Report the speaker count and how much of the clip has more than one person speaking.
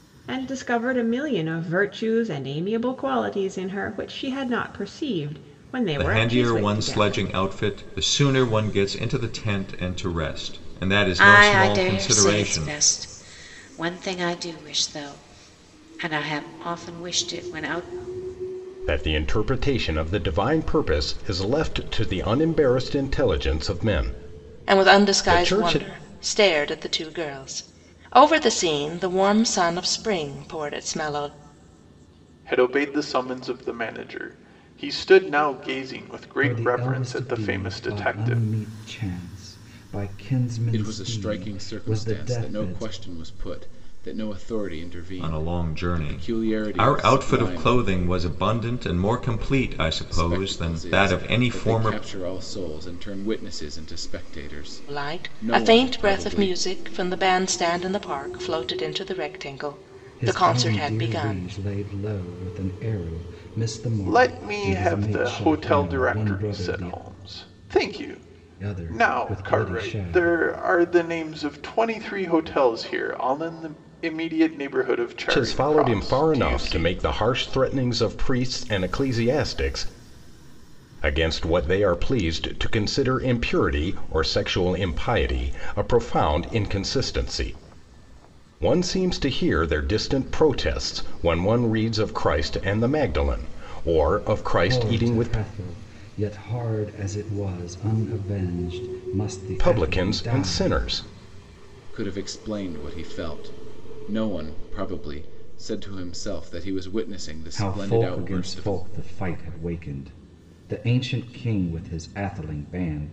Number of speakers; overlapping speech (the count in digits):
8, about 23%